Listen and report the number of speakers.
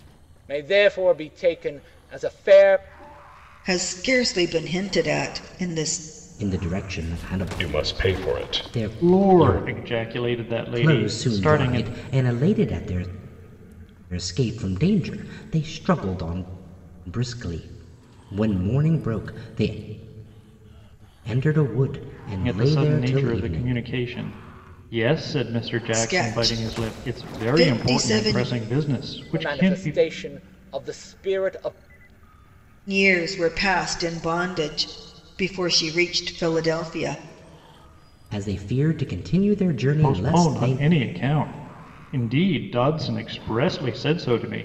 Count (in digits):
5